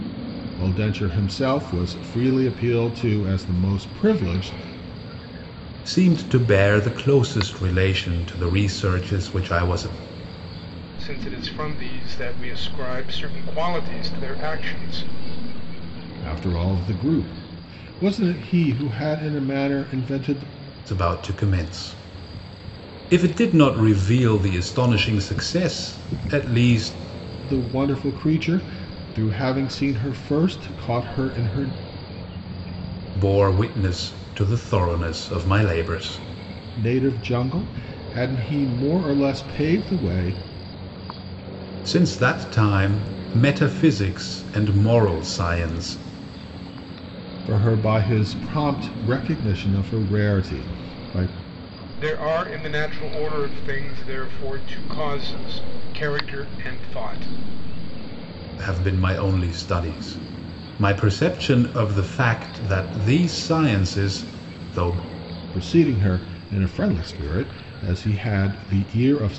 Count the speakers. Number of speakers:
three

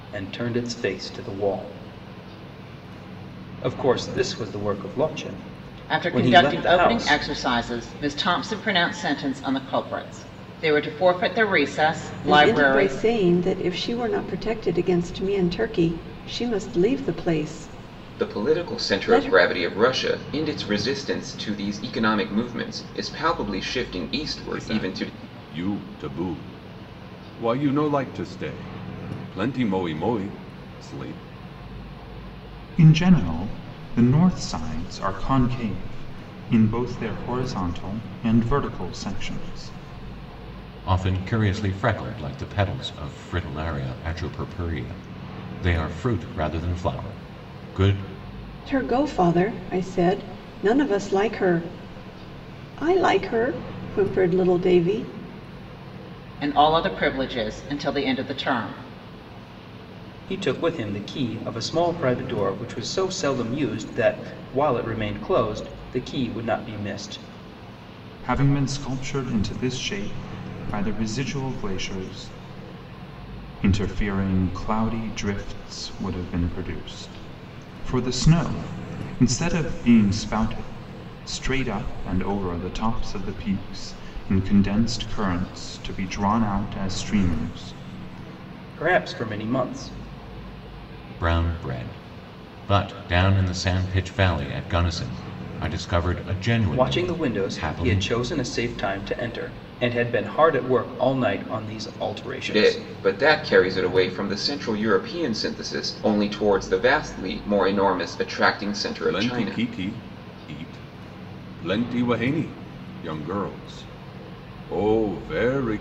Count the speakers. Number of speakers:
seven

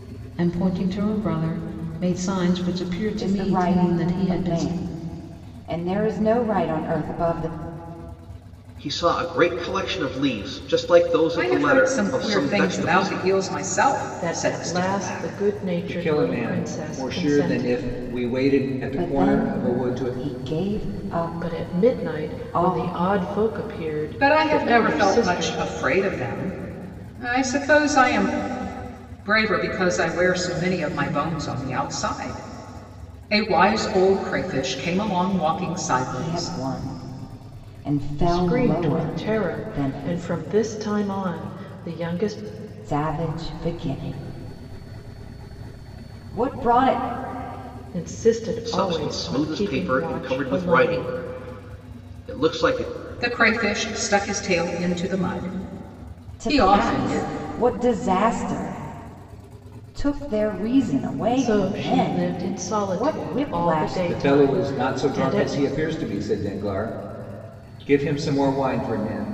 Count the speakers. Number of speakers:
six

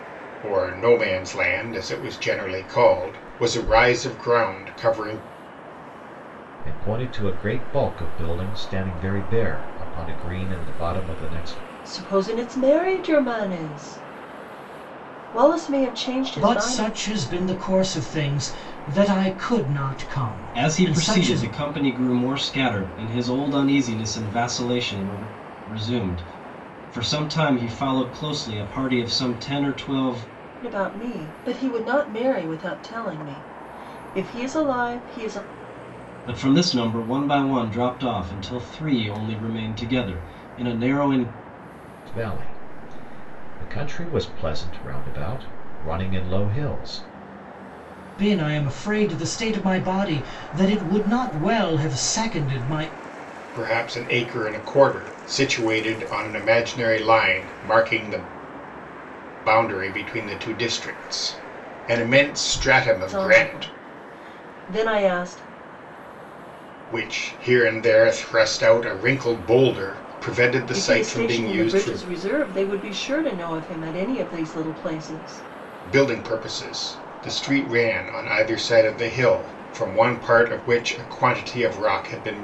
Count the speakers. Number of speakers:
five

